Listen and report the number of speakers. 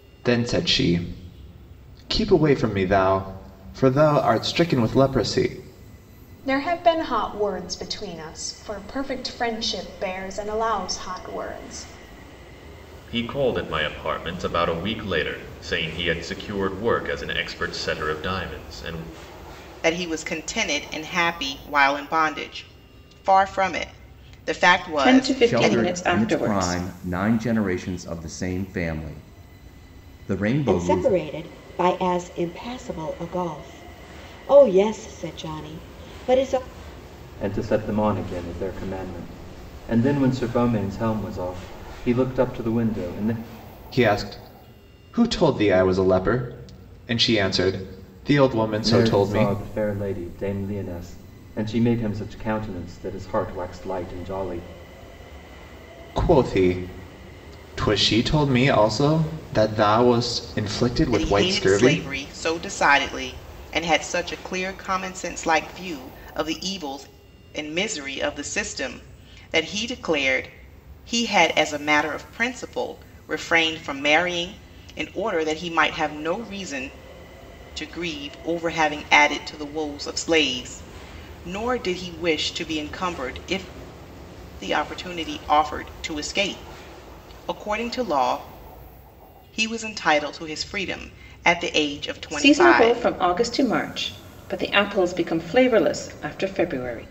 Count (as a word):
eight